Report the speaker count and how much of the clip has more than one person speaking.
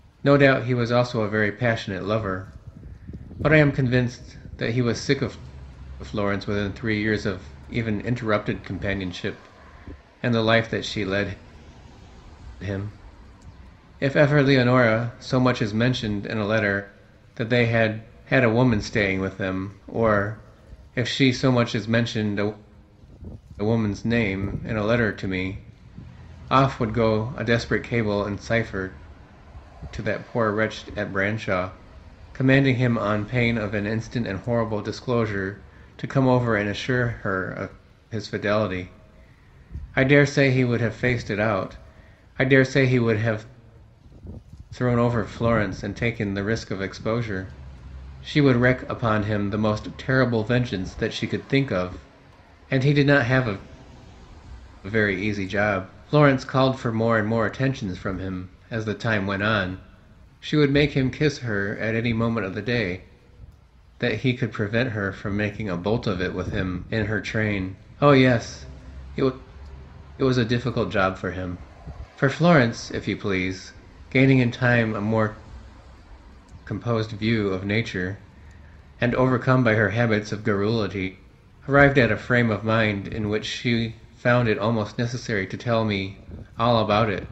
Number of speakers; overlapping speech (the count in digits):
1, no overlap